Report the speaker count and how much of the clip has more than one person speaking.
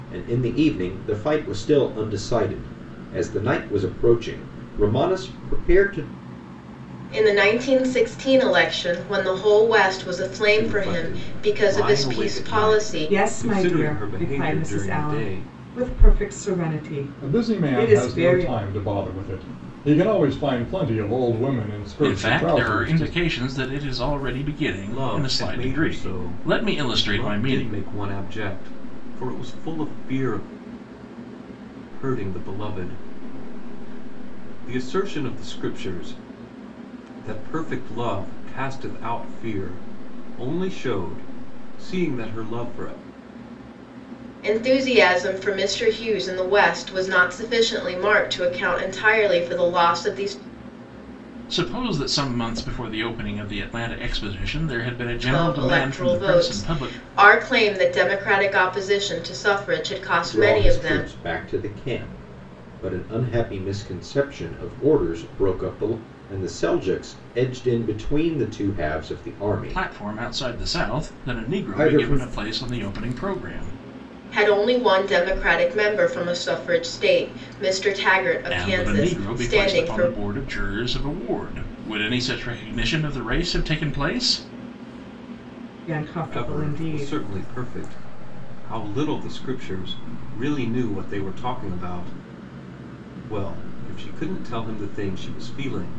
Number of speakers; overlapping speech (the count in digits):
6, about 19%